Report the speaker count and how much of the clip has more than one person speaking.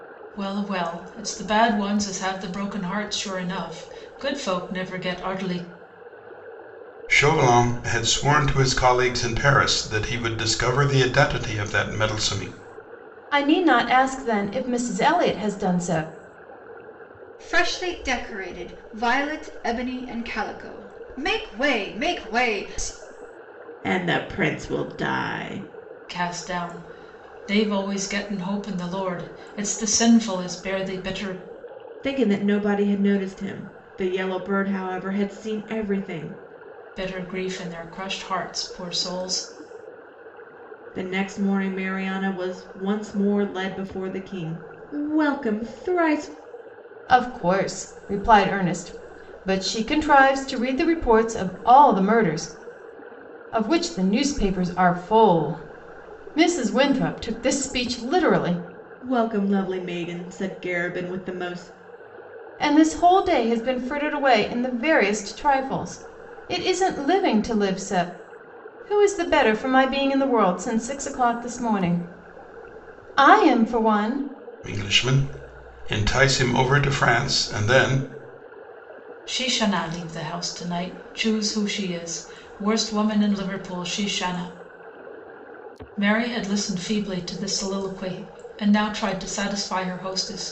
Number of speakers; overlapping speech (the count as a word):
five, no overlap